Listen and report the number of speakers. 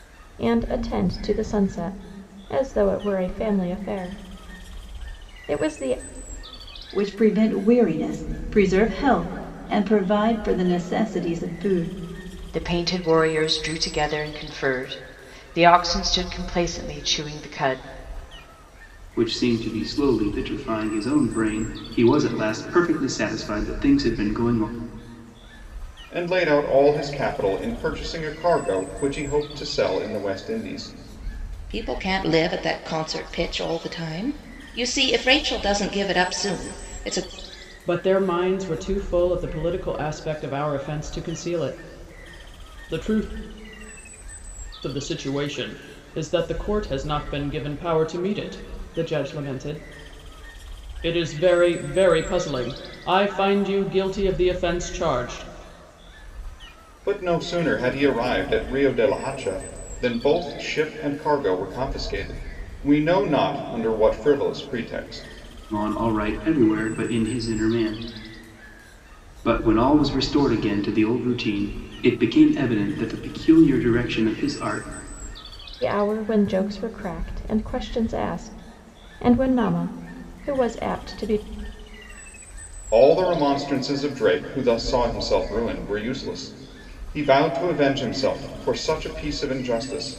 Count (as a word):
seven